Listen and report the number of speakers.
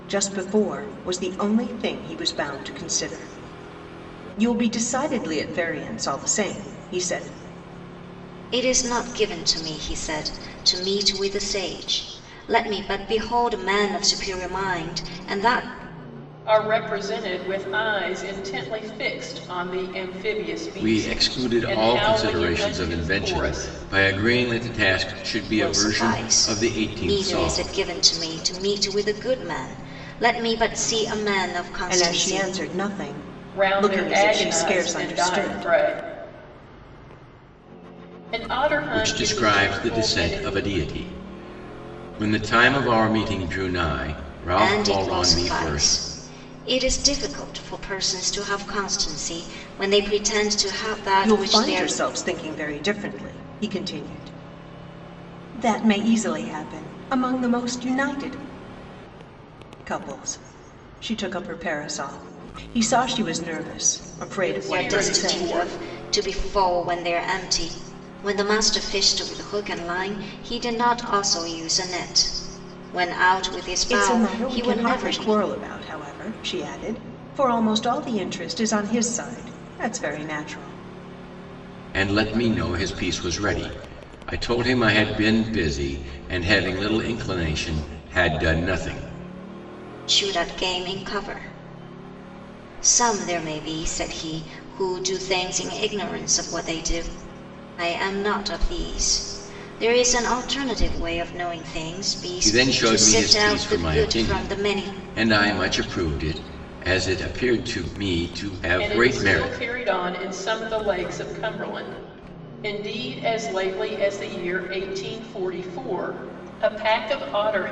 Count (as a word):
four